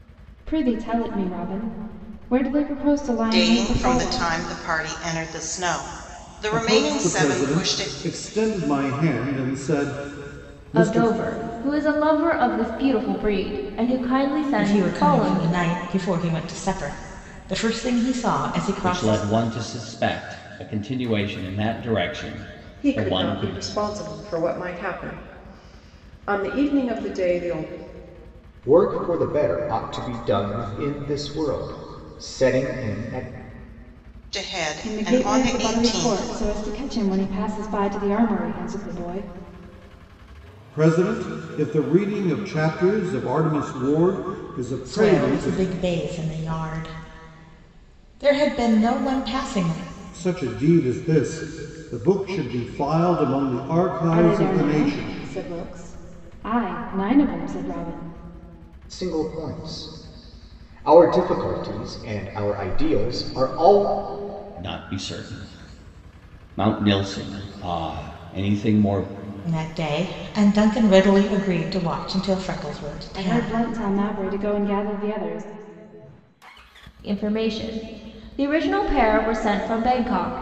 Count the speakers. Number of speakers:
8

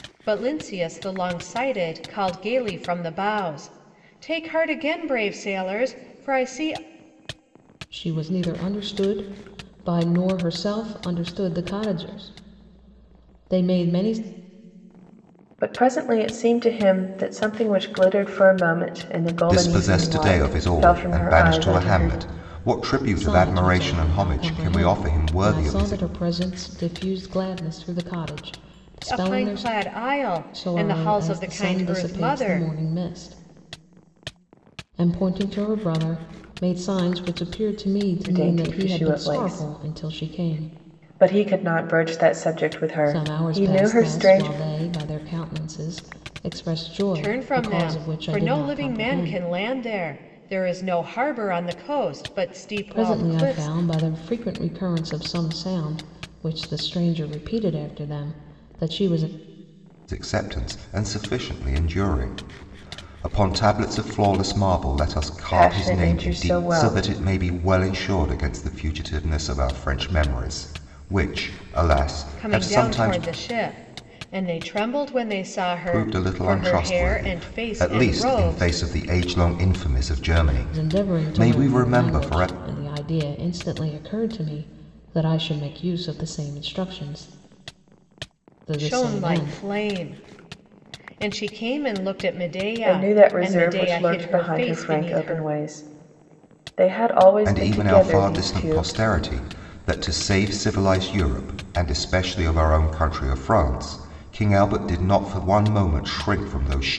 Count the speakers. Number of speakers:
4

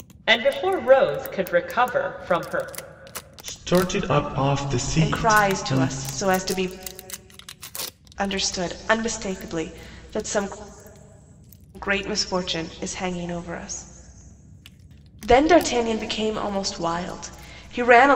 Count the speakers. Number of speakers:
3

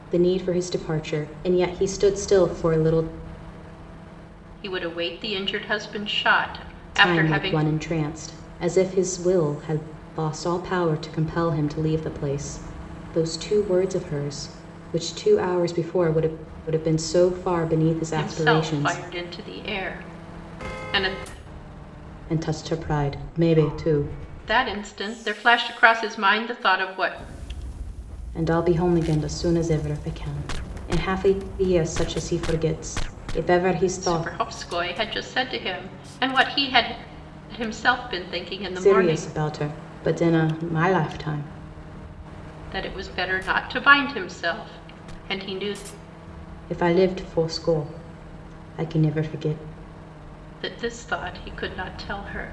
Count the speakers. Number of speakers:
2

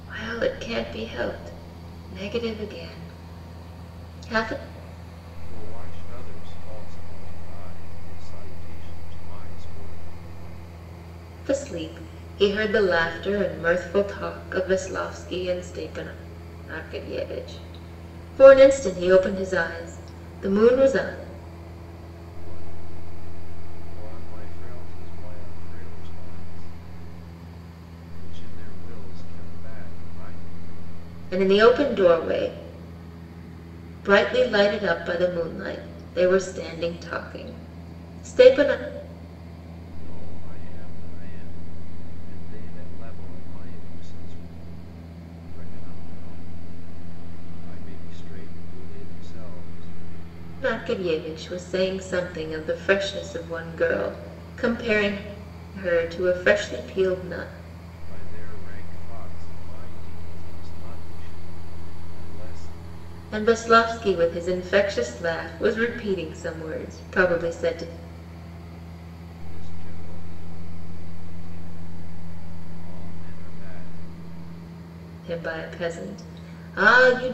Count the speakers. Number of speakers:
2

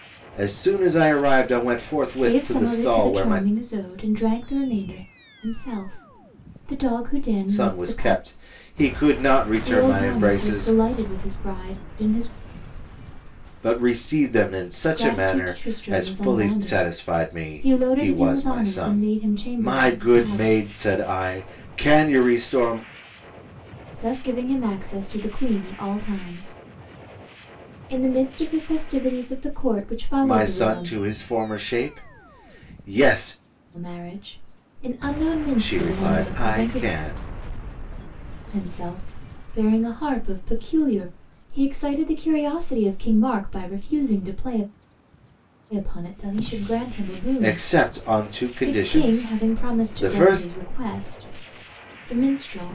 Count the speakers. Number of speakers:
2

